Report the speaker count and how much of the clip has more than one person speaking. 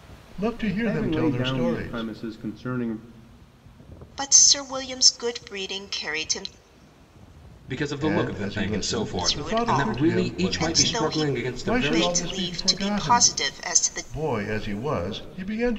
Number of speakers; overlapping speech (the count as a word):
four, about 47%